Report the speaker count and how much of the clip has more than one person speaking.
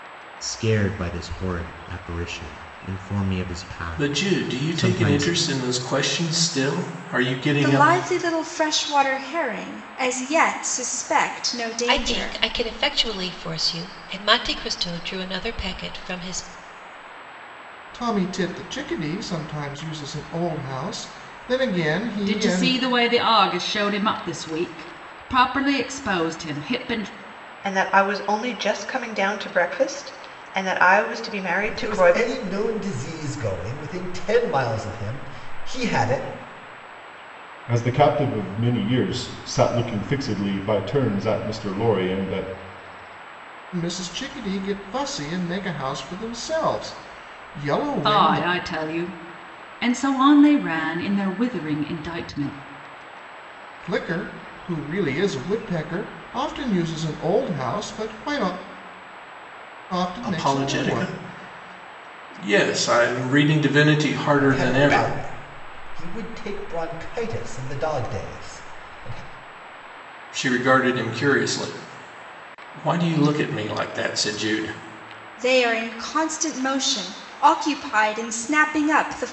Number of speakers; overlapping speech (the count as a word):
nine, about 7%